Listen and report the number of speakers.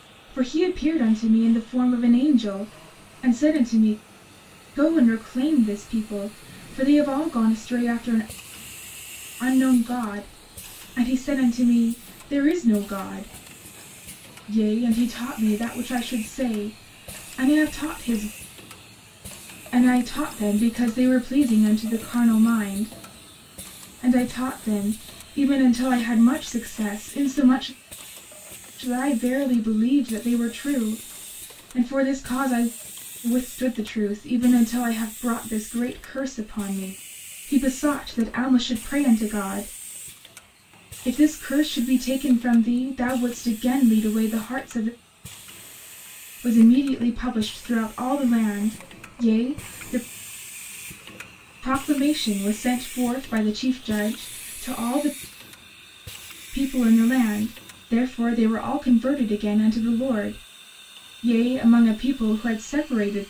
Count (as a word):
one